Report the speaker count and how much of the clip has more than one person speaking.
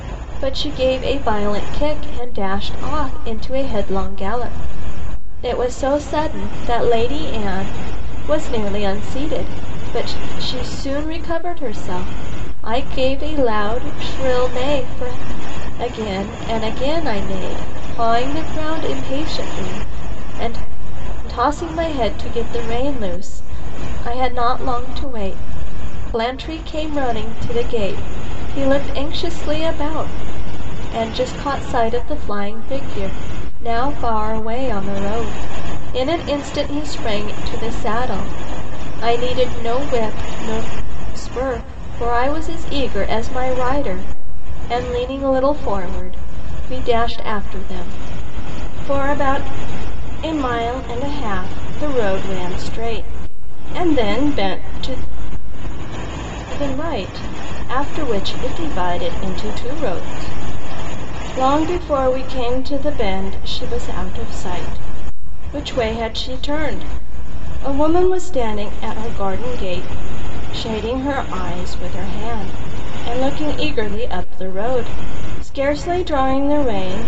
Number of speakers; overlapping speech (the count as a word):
one, no overlap